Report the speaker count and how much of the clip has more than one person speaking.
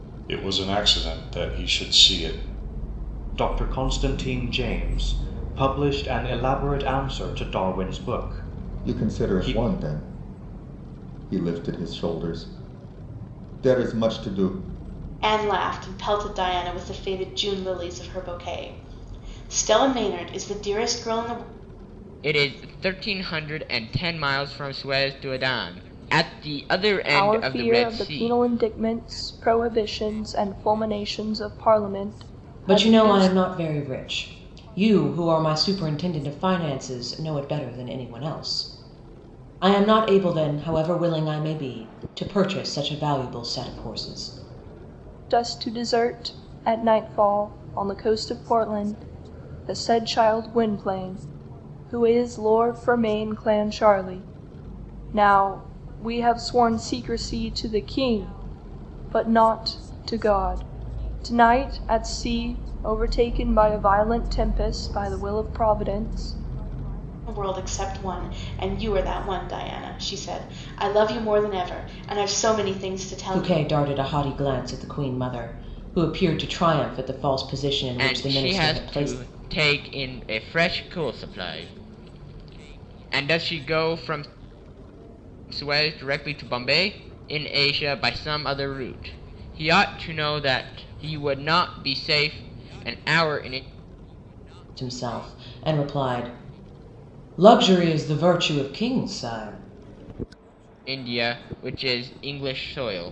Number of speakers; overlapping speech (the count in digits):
7, about 4%